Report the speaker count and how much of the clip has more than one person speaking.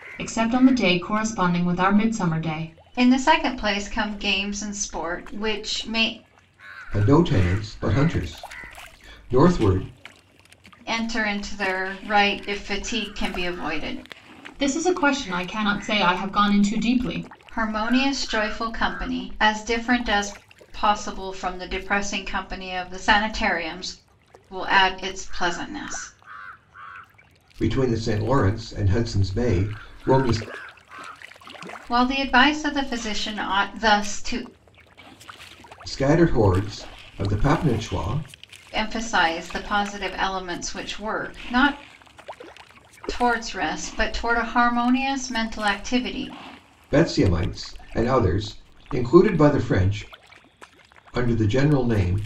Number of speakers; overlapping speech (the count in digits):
3, no overlap